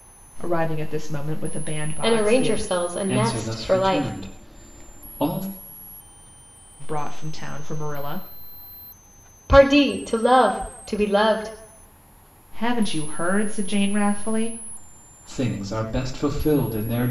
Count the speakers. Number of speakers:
3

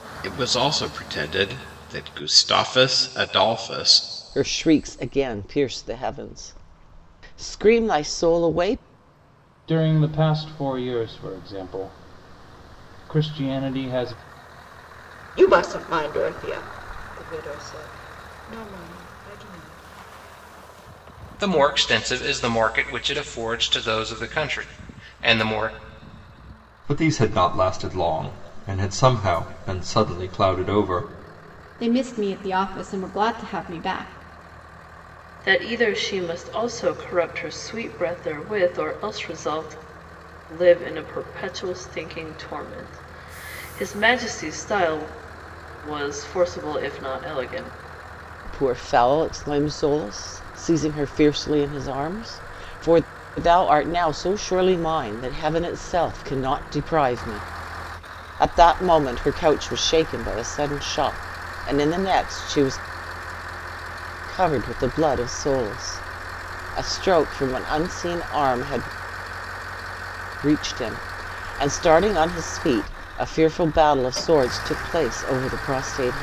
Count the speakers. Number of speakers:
8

